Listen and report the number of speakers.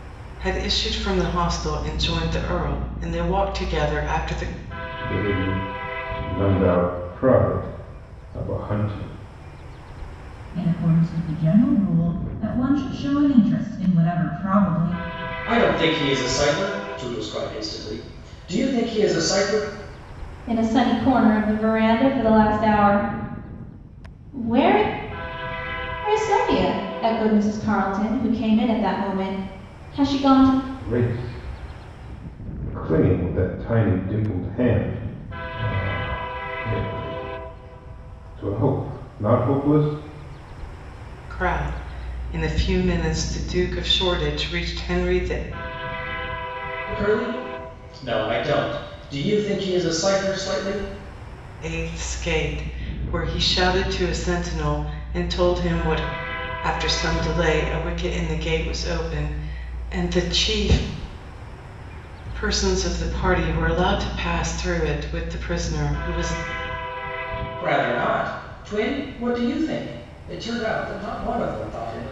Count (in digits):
5